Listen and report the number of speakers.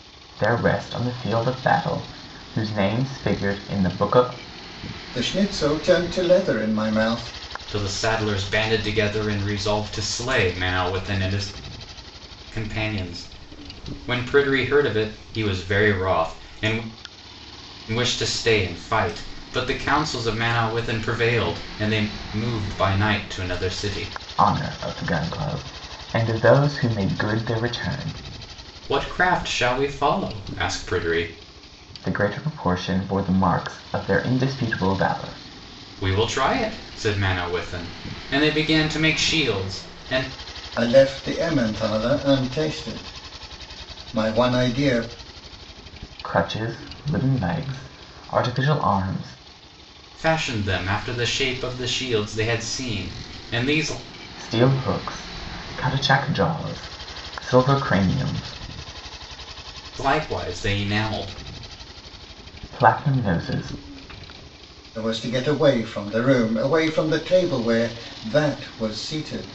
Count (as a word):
three